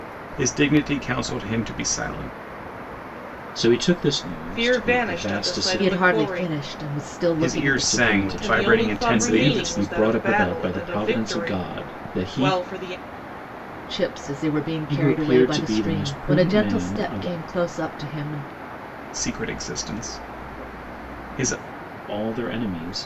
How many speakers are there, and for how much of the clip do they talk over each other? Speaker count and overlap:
four, about 42%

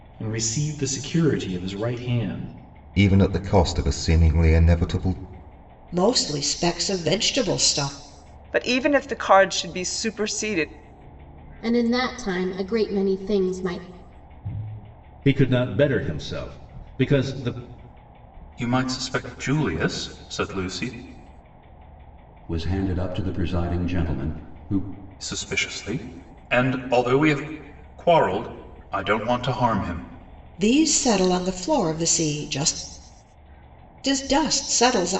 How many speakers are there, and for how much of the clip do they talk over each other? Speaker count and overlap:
eight, no overlap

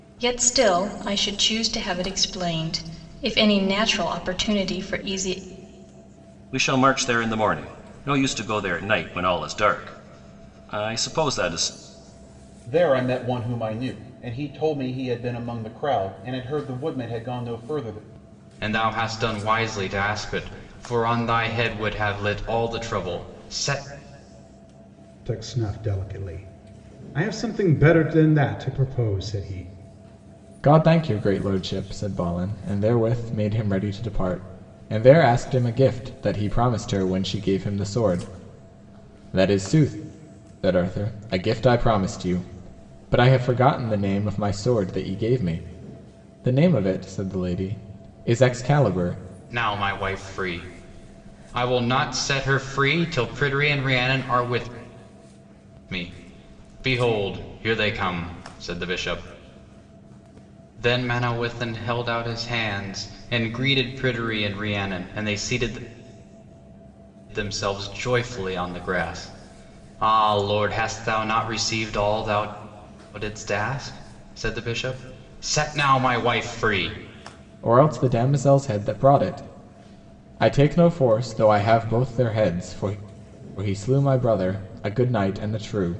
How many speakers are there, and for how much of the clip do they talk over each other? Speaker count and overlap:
six, no overlap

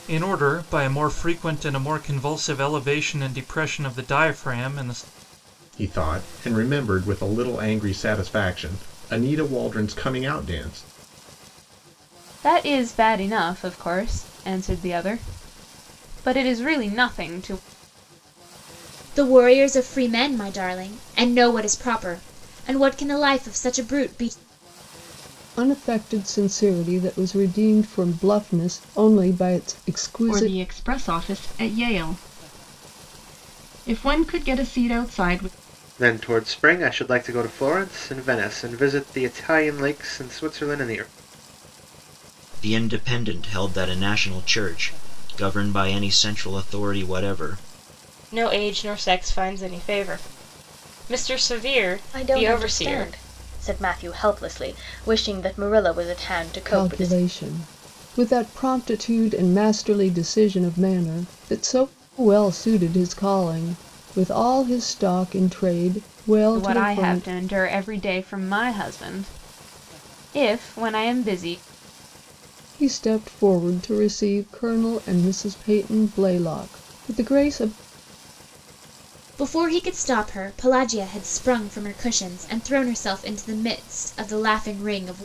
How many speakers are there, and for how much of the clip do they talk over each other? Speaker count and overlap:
ten, about 3%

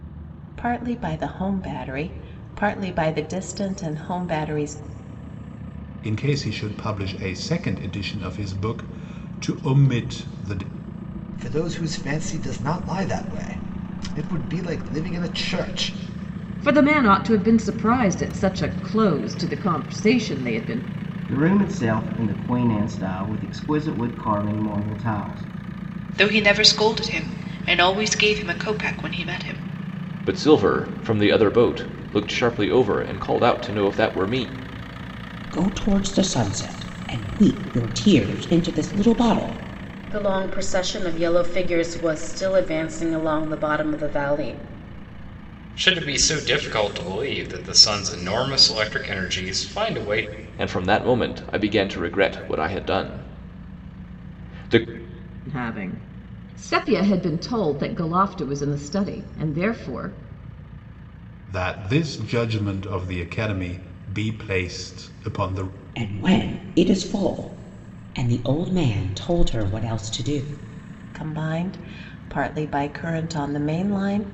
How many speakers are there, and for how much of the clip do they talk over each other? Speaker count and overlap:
ten, no overlap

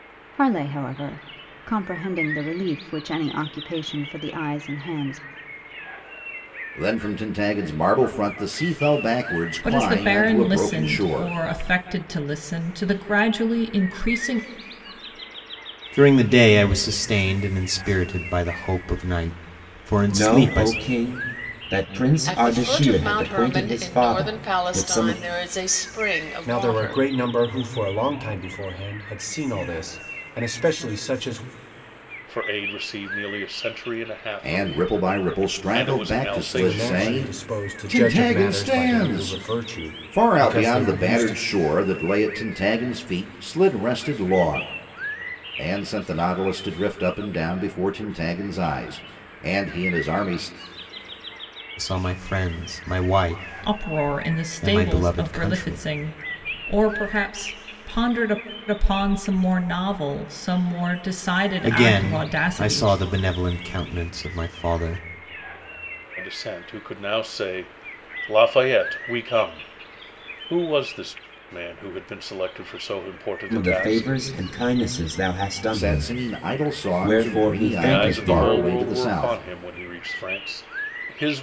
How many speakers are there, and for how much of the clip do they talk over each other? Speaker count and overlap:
eight, about 25%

